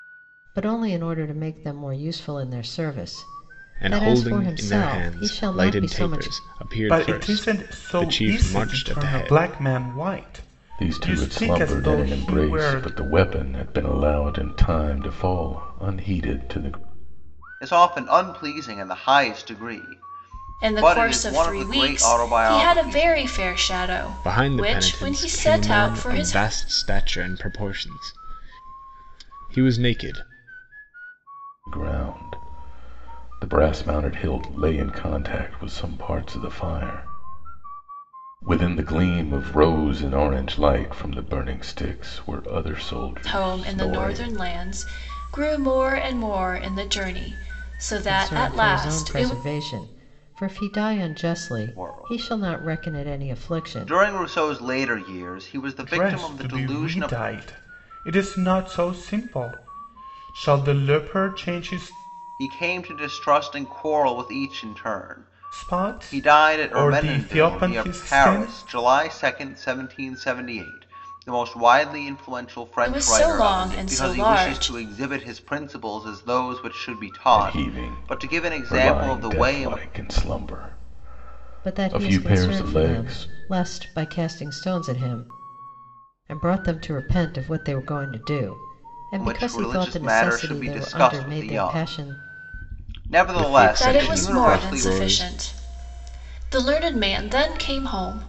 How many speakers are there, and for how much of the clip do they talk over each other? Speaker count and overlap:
6, about 33%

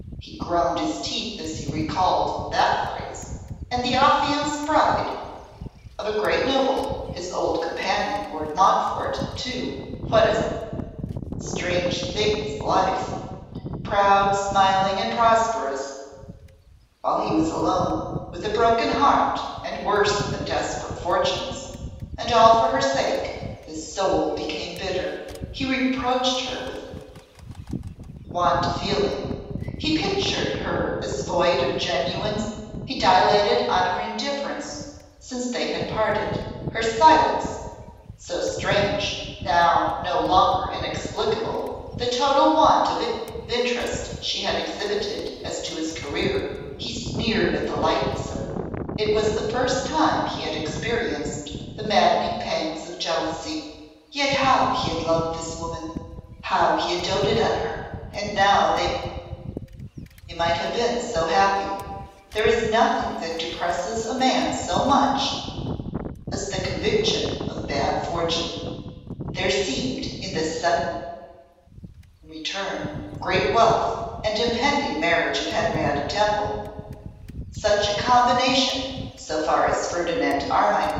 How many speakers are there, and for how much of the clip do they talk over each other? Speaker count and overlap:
1, no overlap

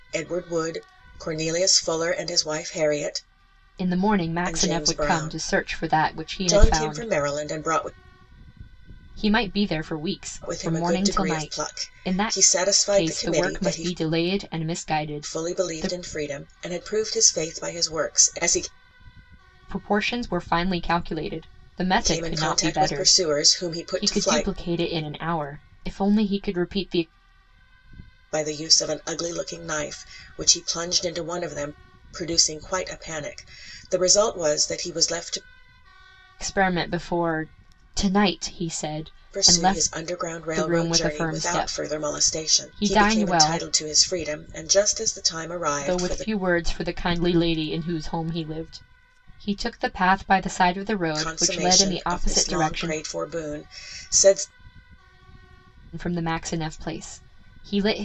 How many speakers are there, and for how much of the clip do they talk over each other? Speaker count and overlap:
2, about 25%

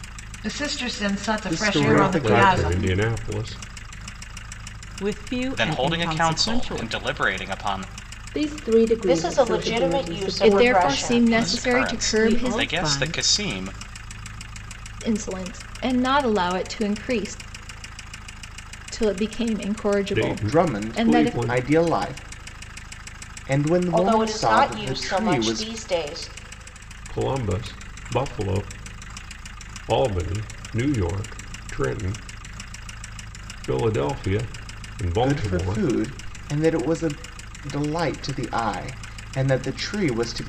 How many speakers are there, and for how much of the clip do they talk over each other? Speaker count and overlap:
8, about 28%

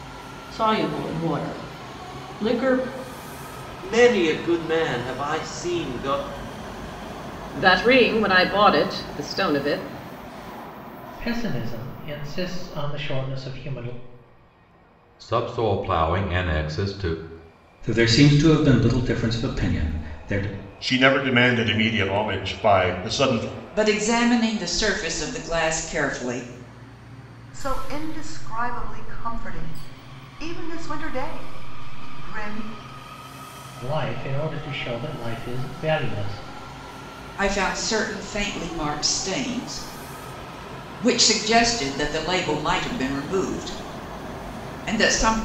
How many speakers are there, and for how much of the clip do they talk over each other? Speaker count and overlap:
9, no overlap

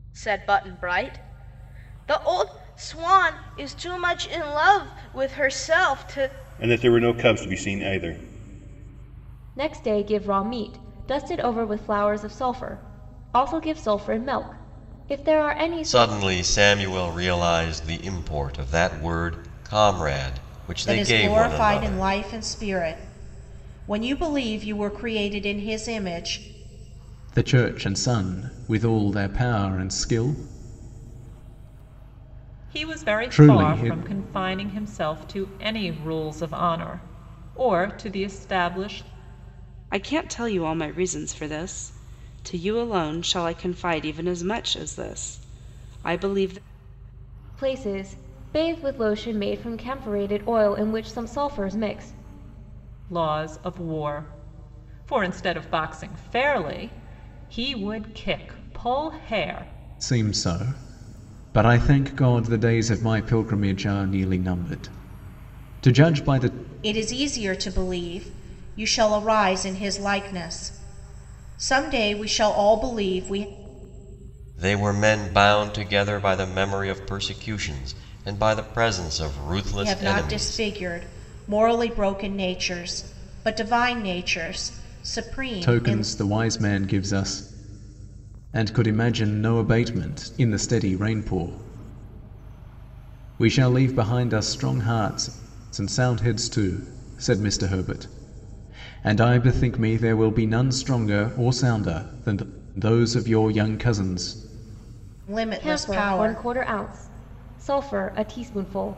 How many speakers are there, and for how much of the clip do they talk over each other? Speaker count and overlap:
8, about 5%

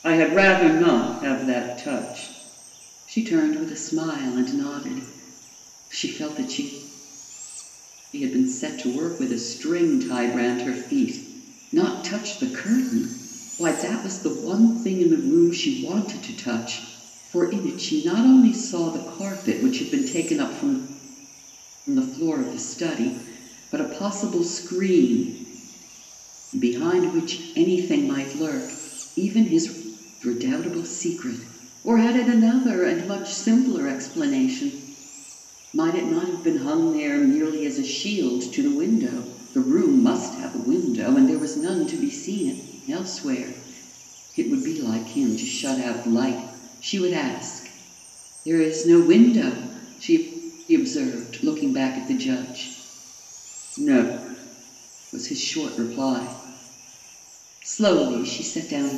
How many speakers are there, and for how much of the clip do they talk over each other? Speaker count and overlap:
1, no overlap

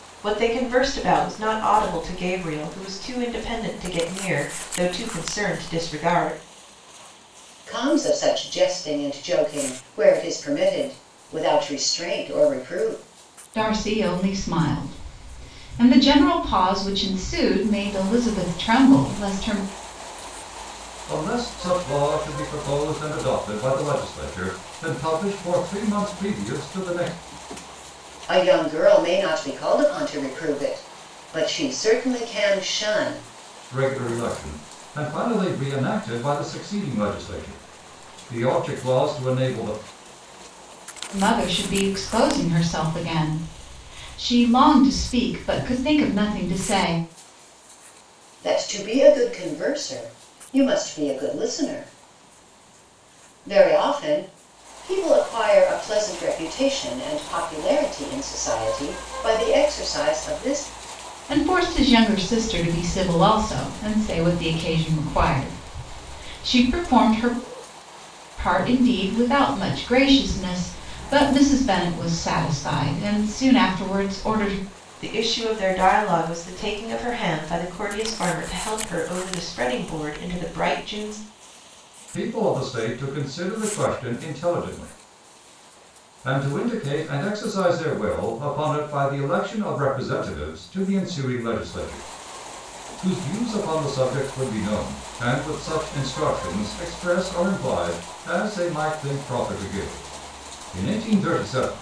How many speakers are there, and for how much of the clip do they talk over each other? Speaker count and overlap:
4, no overlap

